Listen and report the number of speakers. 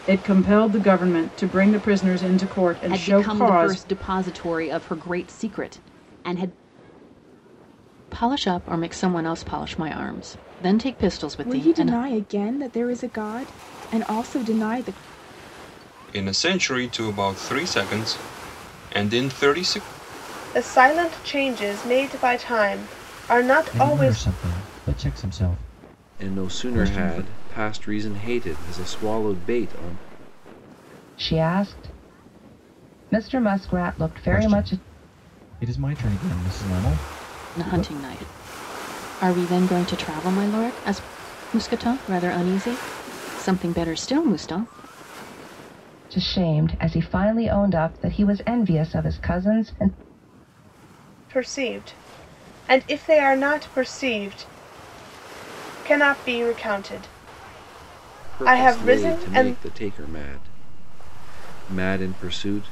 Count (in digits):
9